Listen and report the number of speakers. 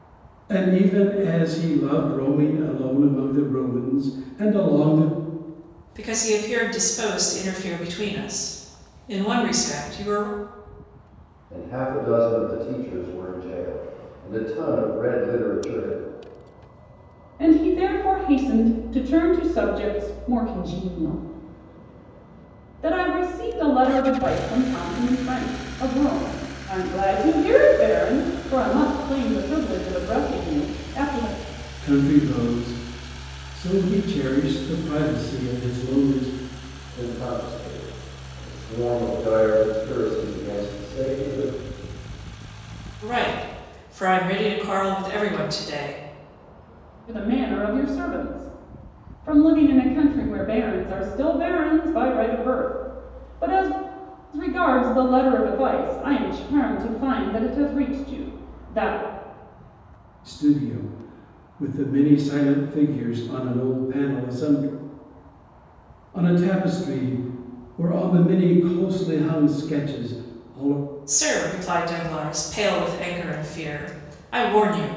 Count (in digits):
4